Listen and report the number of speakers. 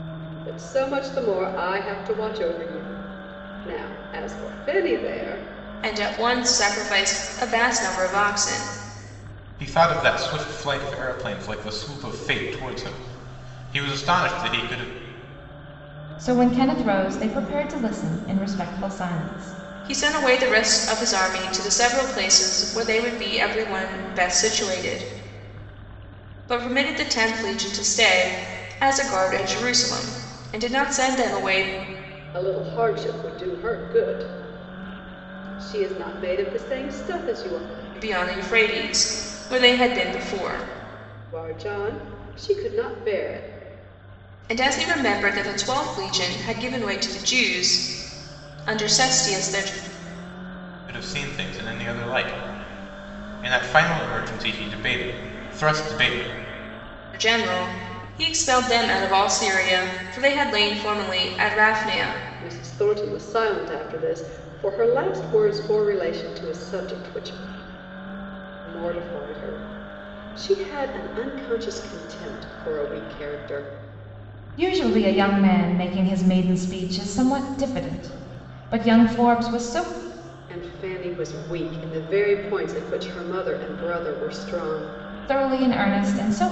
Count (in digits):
4